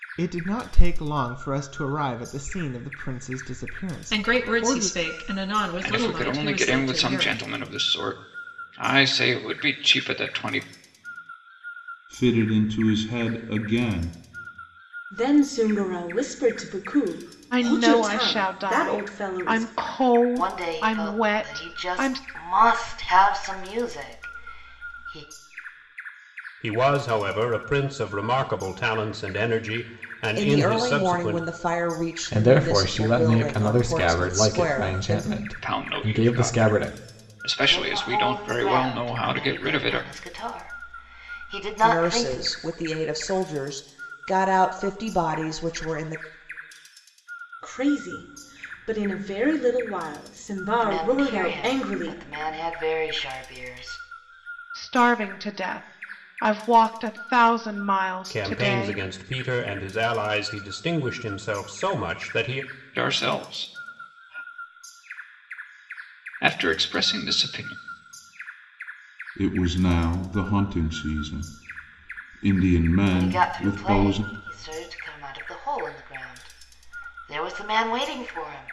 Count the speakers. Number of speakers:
10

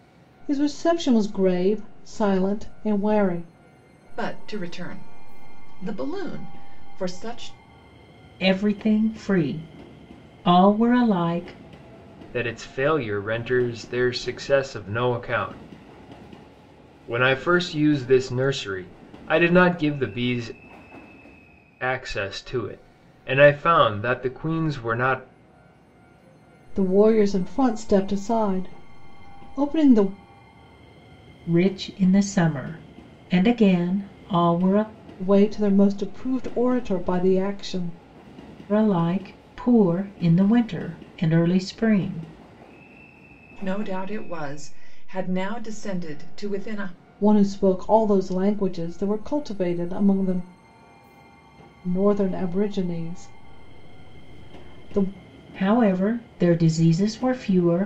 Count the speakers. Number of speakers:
4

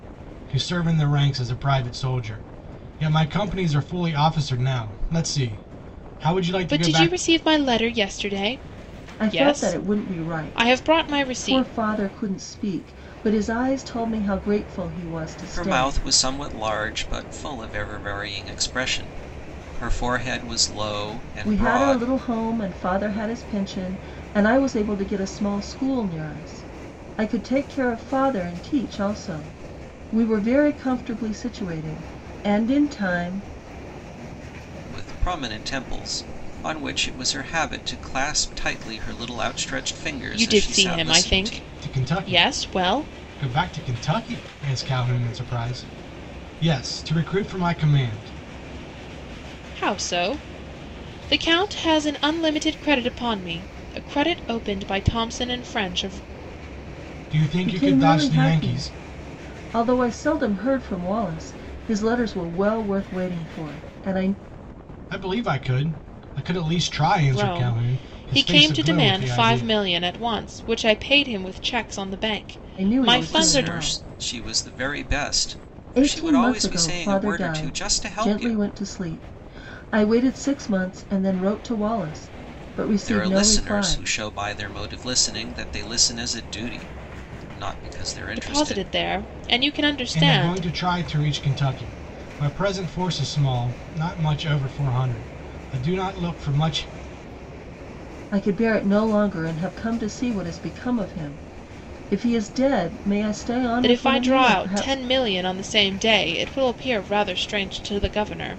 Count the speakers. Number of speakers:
4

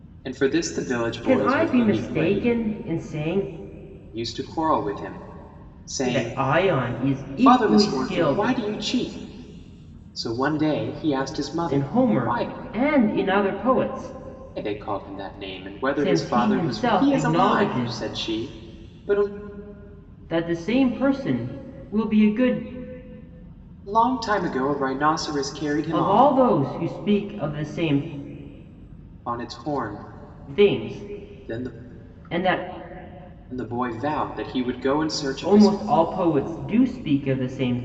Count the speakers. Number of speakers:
2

